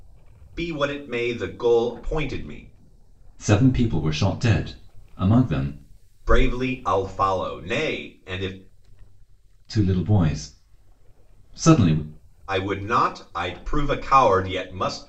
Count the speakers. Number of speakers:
2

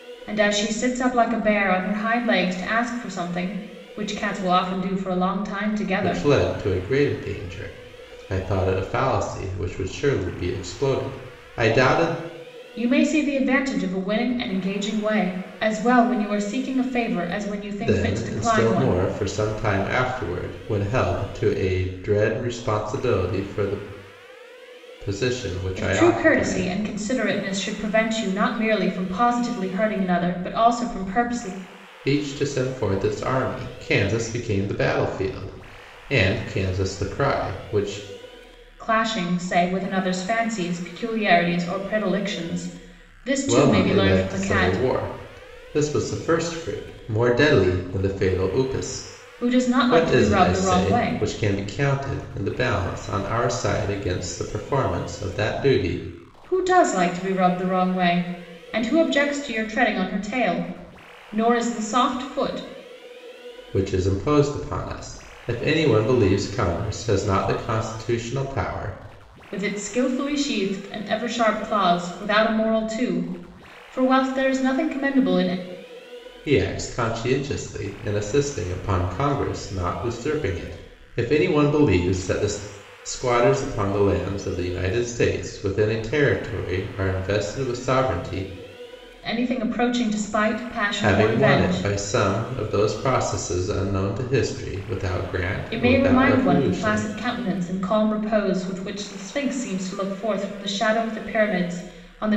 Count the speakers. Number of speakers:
2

